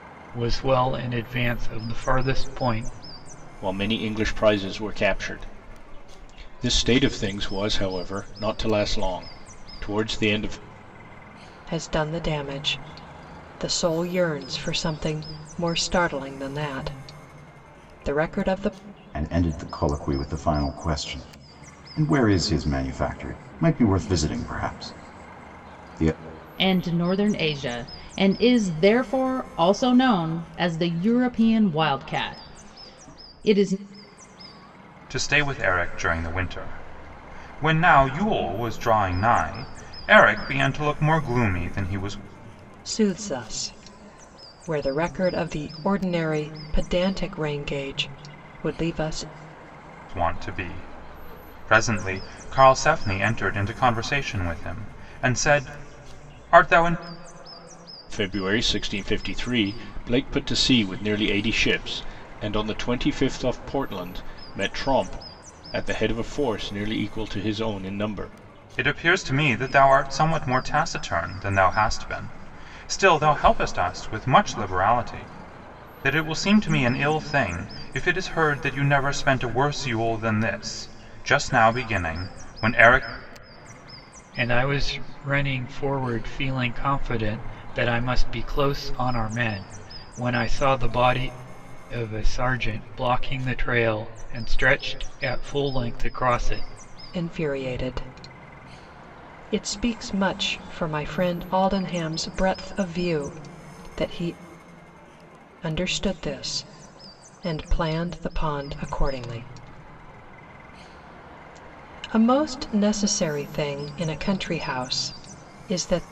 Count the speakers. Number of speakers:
6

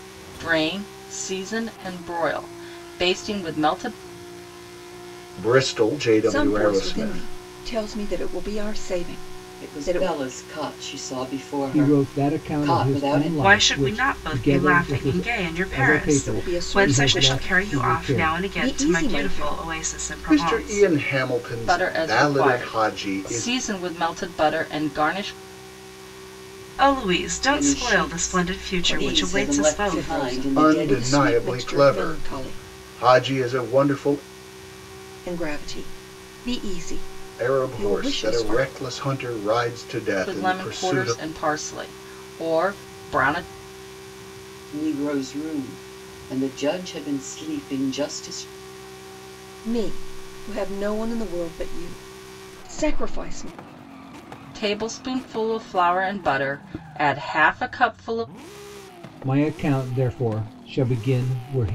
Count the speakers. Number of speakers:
6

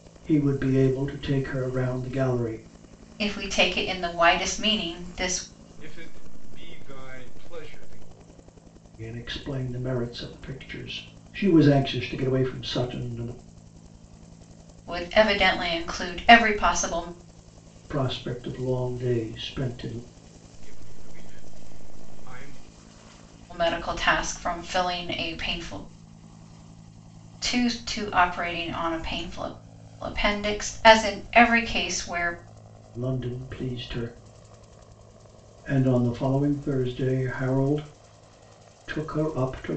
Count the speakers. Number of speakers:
3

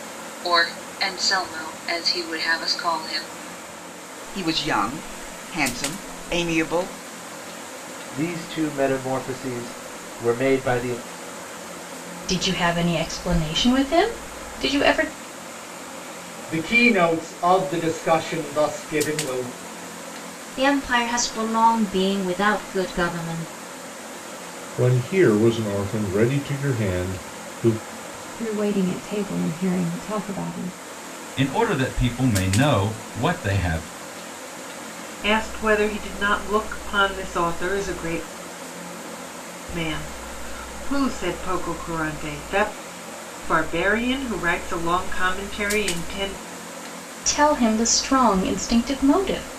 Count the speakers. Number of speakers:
10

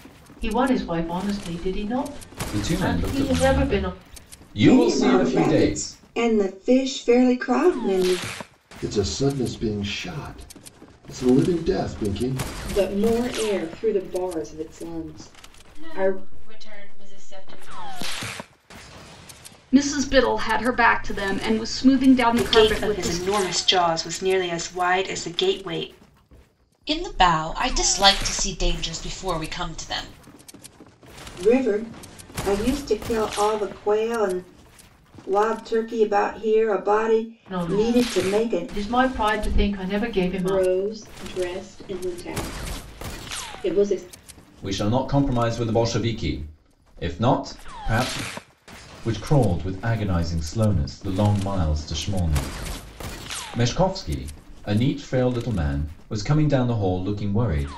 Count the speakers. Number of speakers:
9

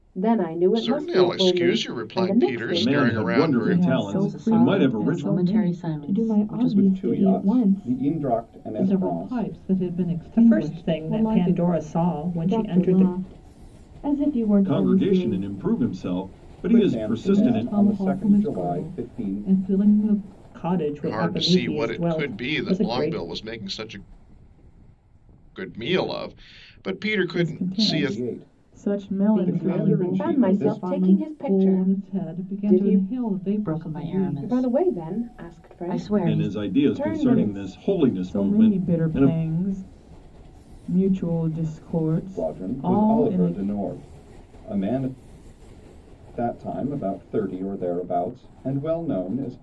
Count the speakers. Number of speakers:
9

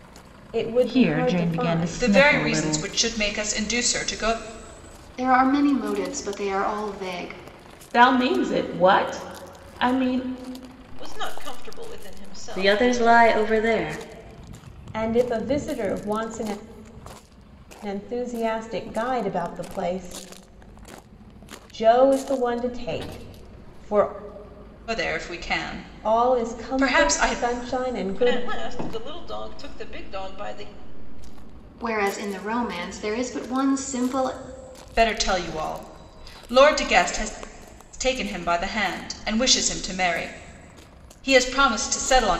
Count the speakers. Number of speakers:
7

